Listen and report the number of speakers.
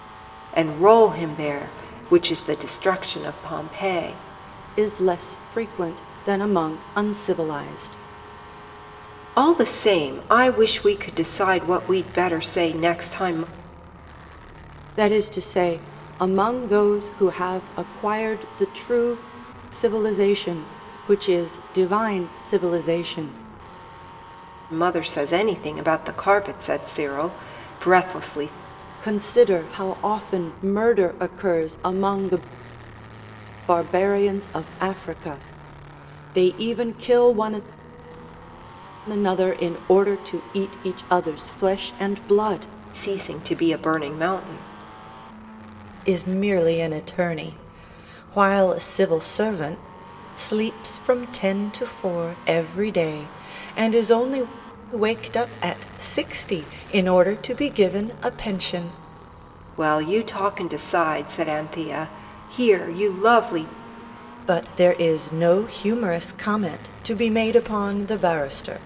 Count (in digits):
2